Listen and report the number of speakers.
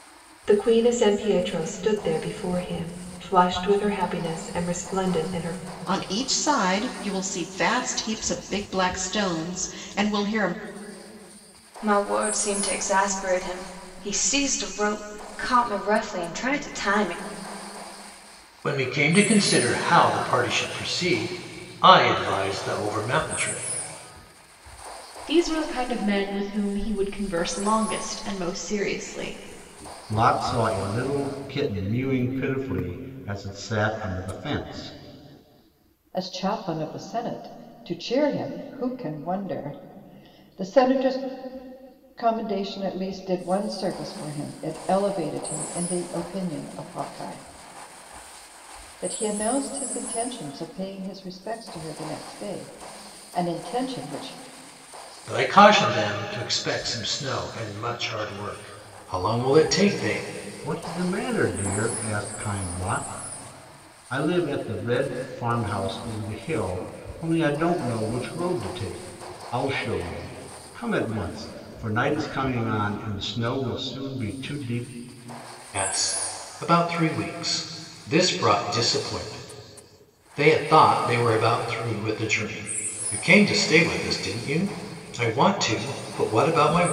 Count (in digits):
7